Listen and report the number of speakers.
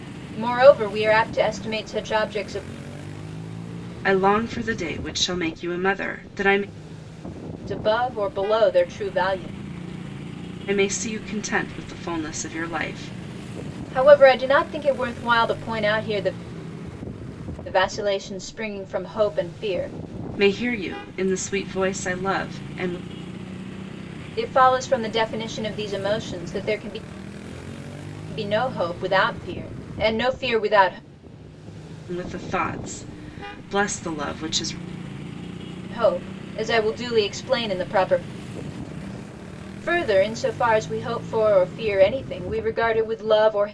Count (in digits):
2